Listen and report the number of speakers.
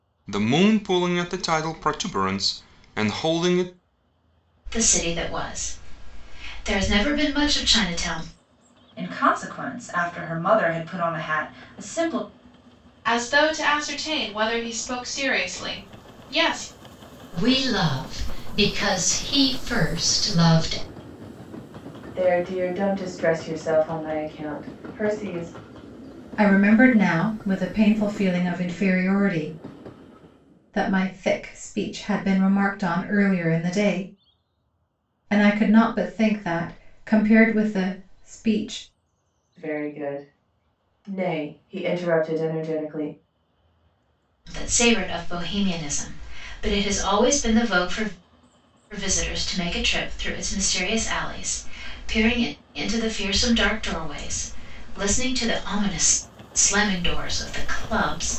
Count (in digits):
7